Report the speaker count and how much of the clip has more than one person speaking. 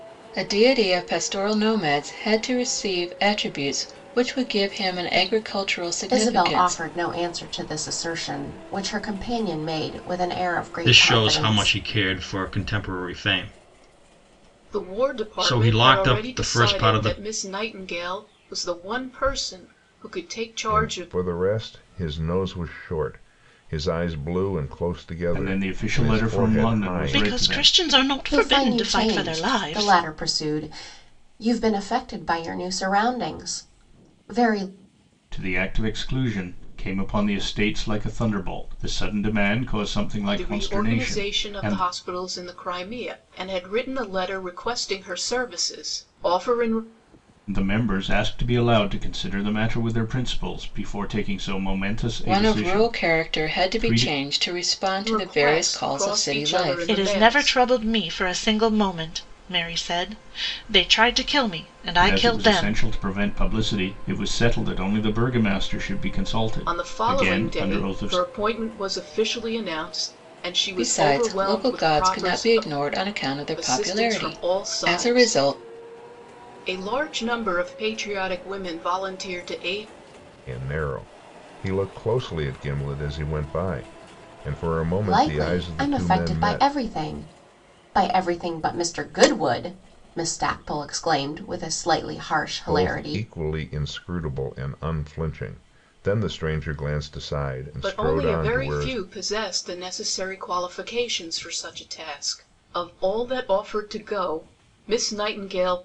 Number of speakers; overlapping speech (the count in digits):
7, about 24%